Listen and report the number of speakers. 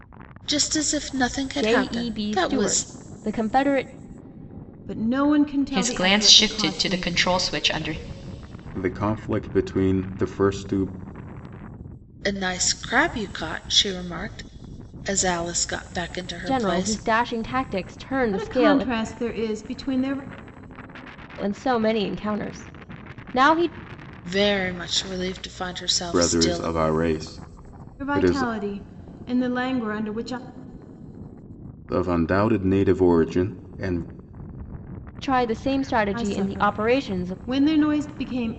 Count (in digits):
5